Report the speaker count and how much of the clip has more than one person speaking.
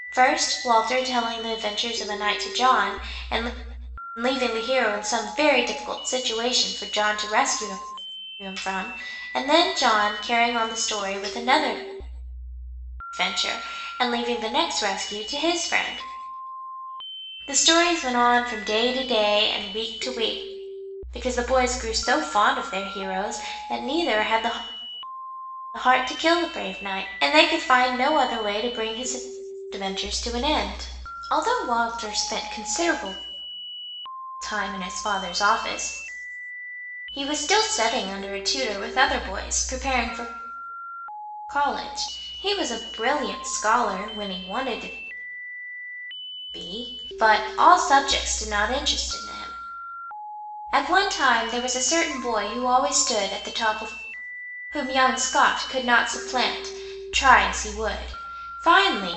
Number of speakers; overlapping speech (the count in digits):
1, no overlap